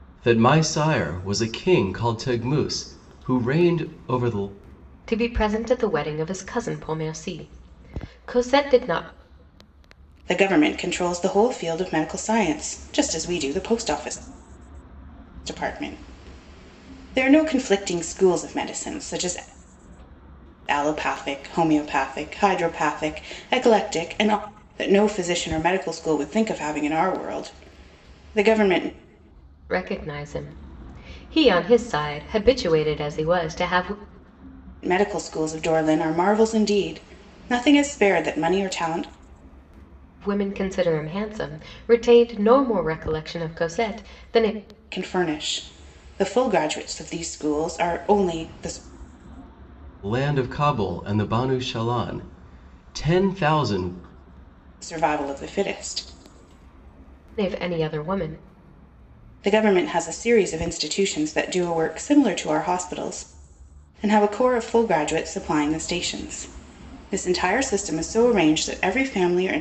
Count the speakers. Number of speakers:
3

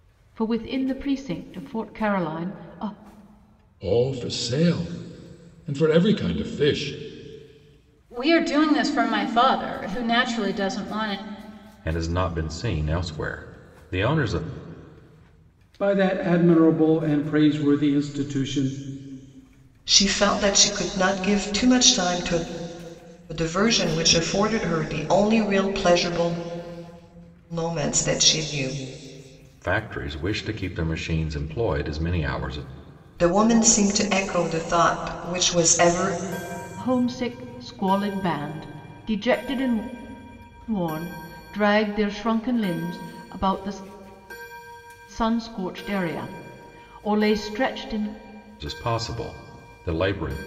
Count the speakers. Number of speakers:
6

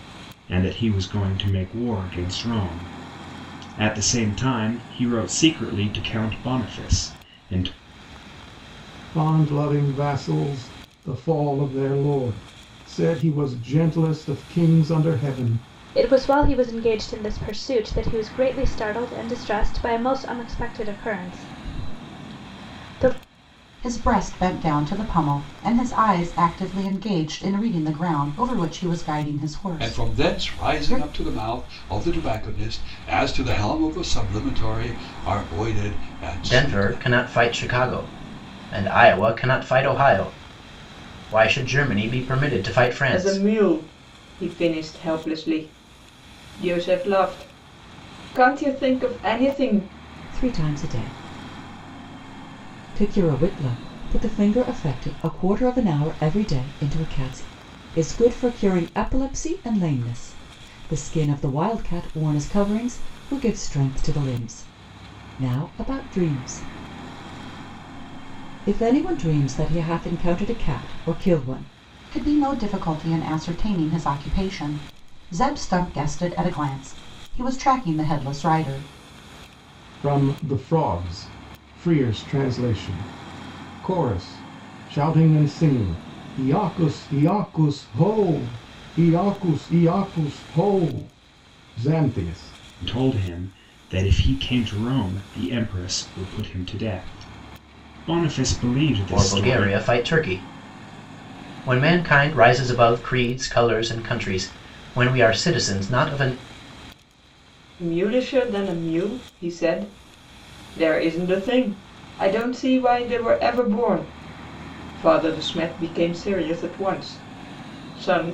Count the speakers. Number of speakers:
8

